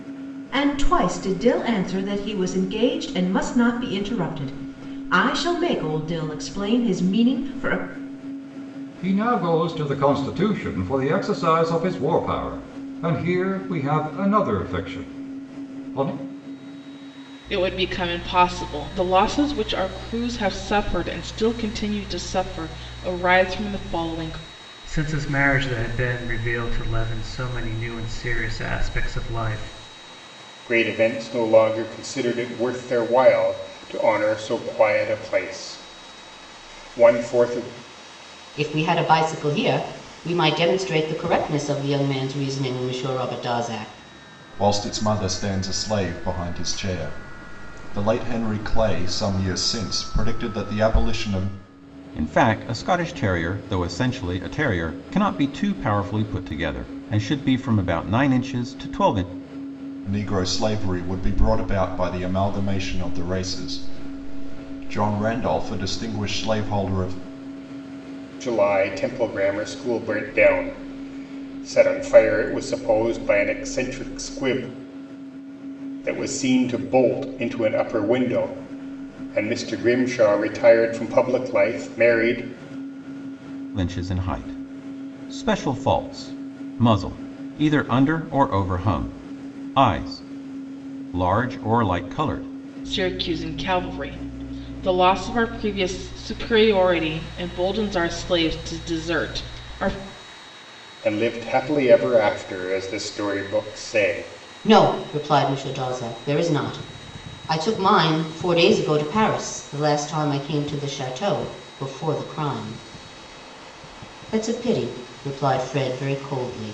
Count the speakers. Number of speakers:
8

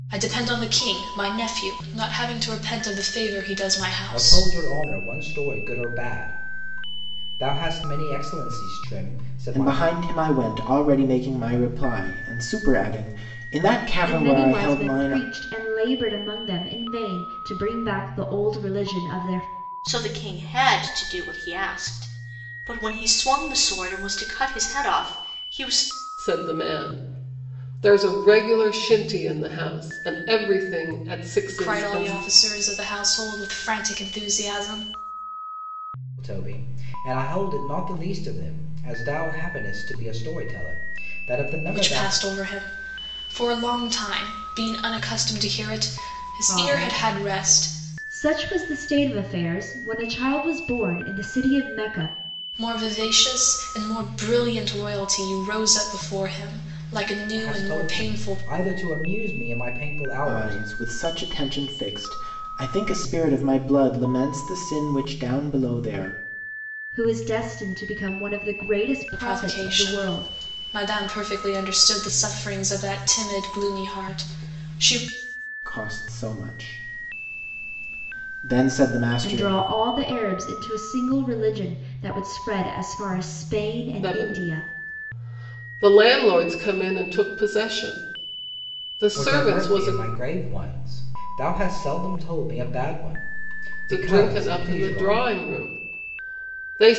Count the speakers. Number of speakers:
6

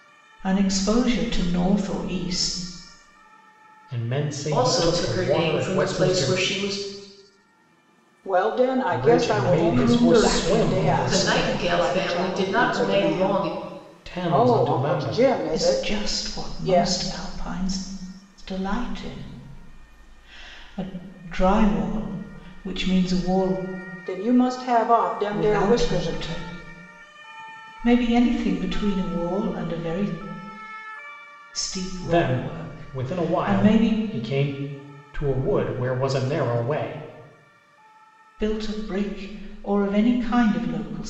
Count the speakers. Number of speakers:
4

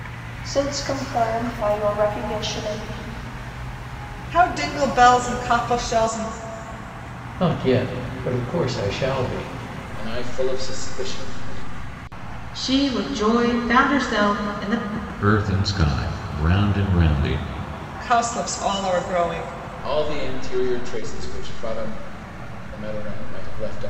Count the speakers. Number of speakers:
6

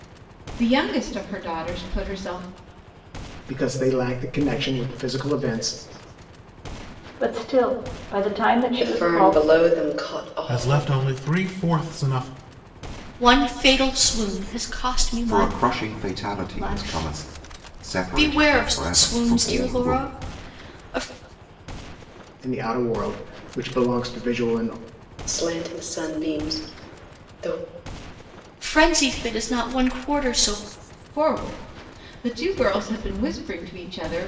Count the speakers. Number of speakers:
7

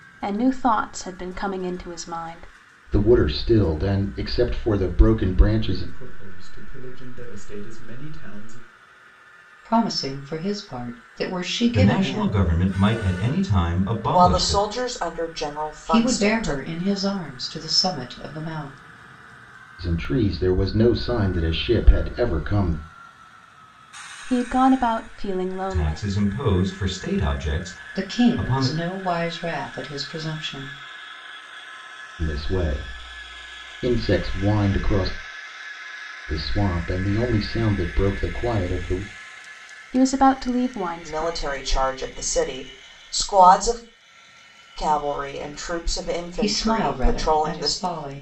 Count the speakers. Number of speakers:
6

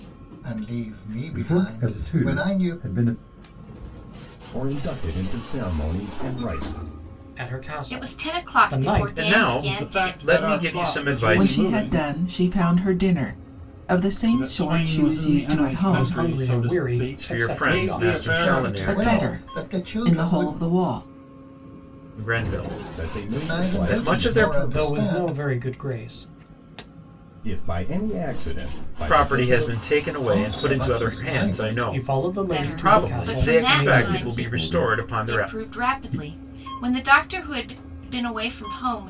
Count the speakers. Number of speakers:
8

